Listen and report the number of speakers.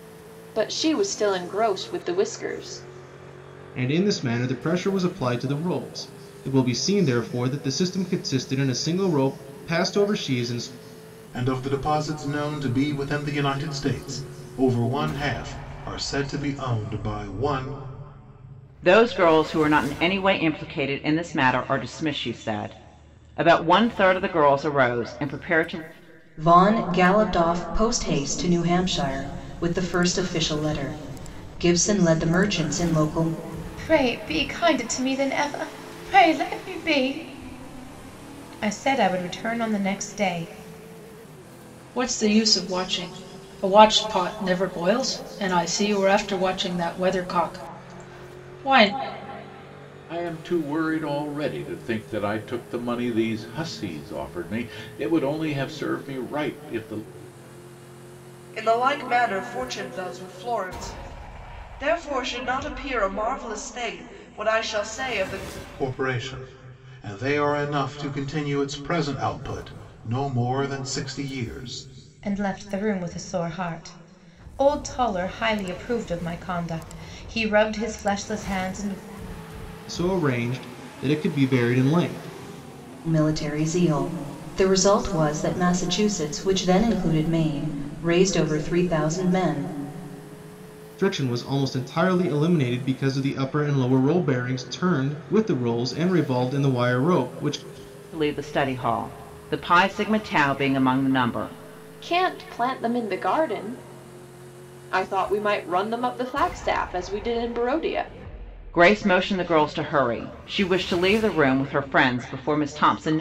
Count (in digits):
9